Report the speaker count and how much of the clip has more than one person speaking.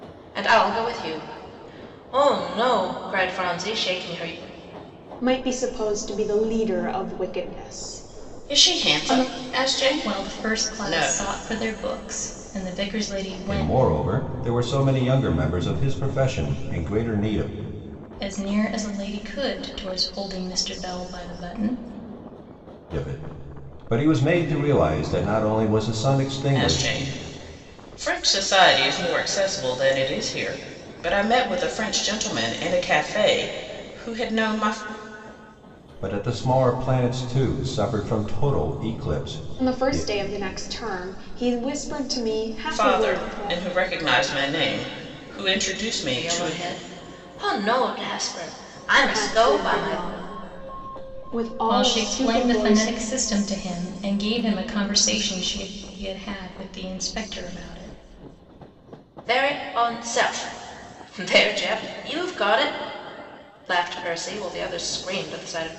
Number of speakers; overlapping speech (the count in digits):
5, about 11%